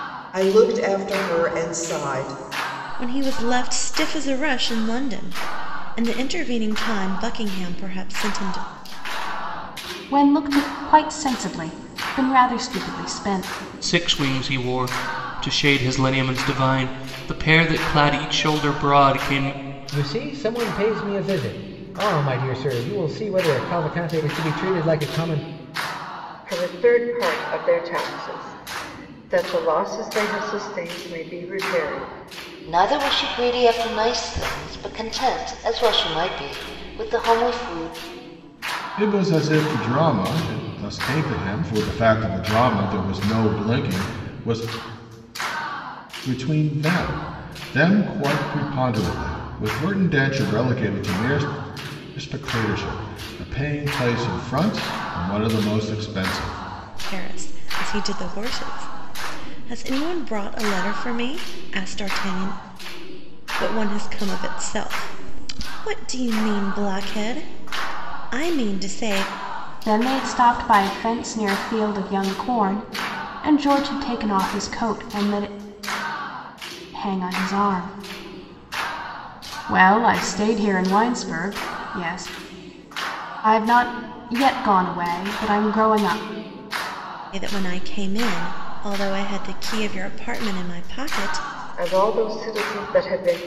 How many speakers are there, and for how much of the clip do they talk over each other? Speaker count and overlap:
8, no overlap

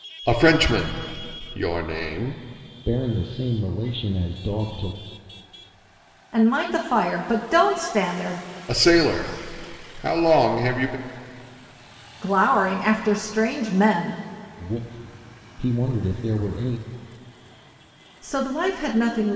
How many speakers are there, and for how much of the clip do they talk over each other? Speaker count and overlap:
3, no overlap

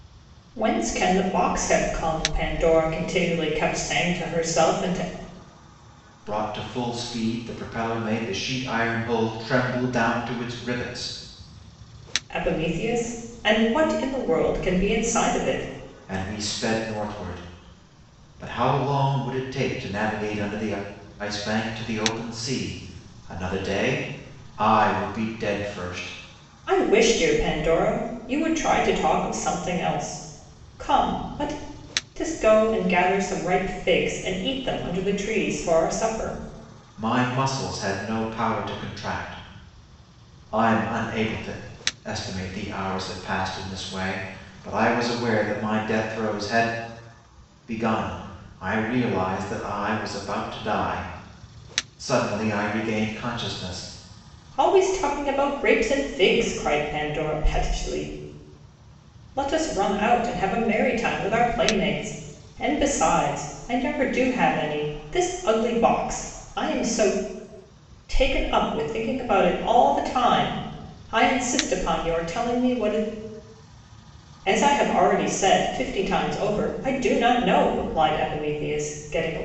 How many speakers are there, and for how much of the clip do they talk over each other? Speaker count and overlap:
2, no overlap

